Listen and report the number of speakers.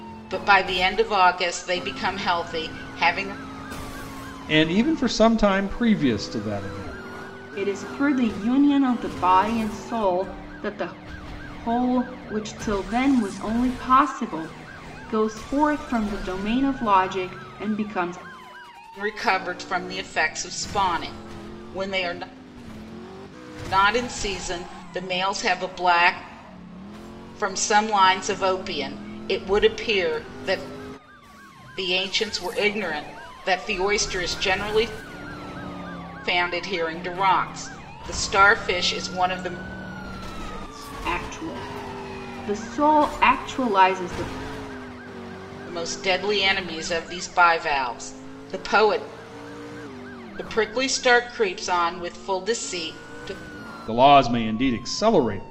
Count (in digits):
3